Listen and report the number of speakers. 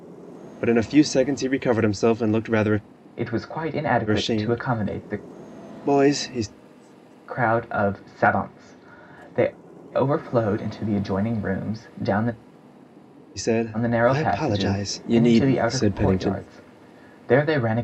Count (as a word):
two